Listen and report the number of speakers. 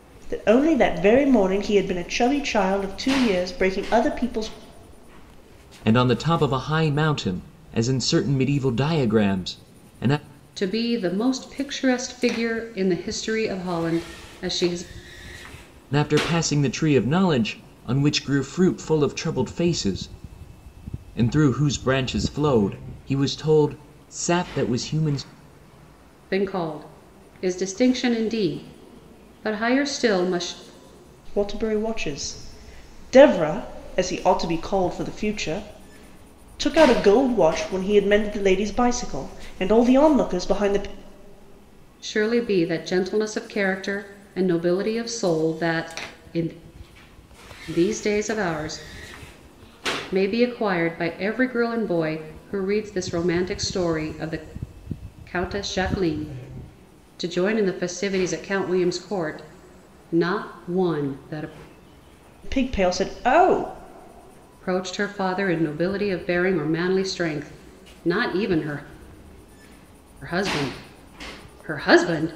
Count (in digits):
3